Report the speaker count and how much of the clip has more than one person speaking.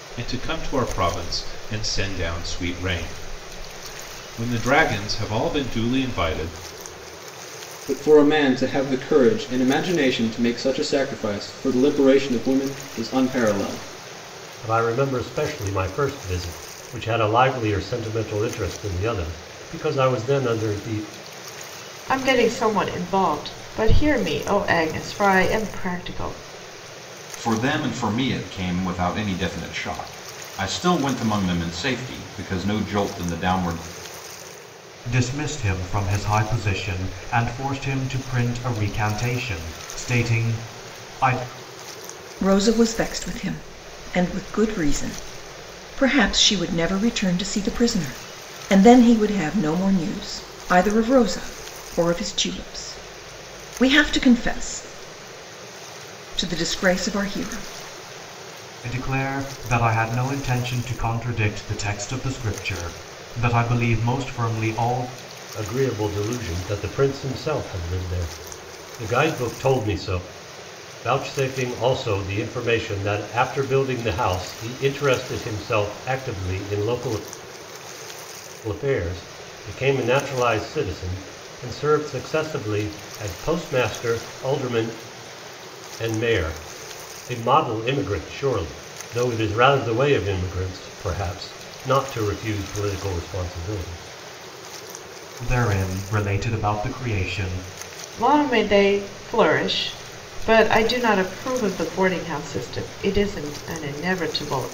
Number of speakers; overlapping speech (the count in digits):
7, no overlap